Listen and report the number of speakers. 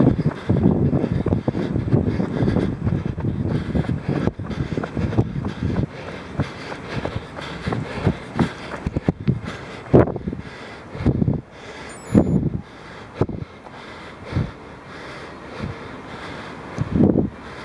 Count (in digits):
0